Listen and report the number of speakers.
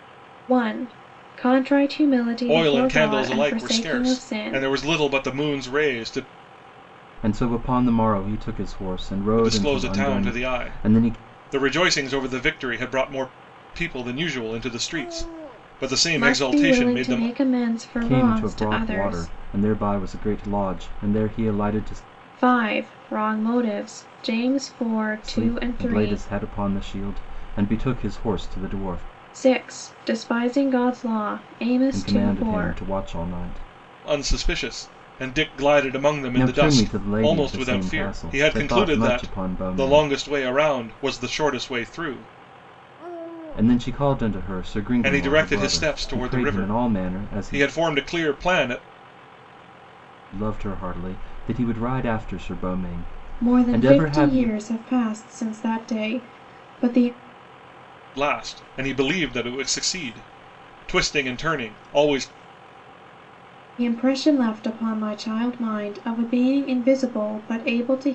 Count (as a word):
three